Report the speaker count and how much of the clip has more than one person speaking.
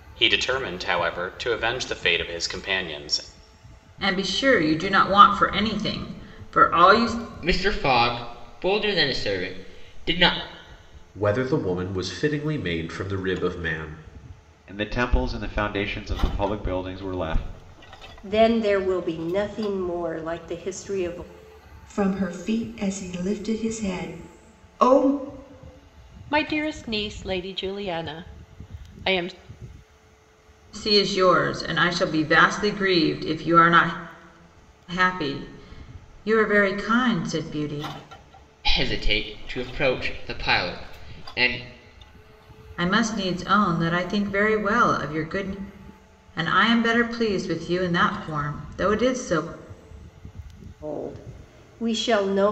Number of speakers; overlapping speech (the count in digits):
8, no overlap